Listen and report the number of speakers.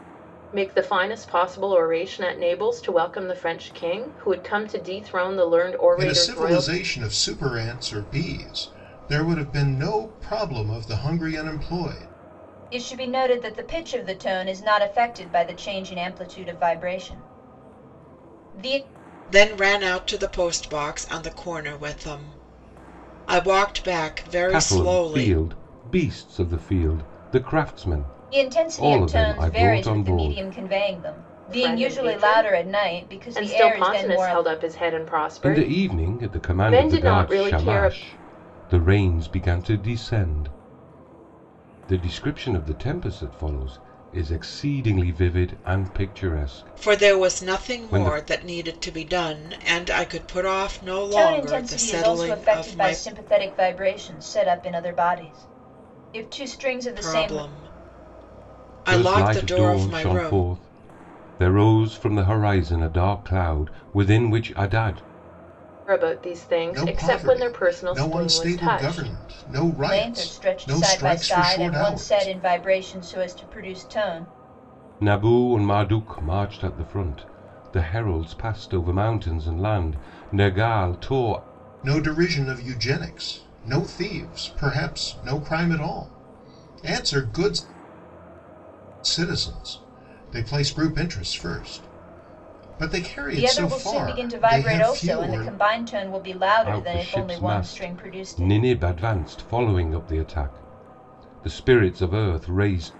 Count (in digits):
5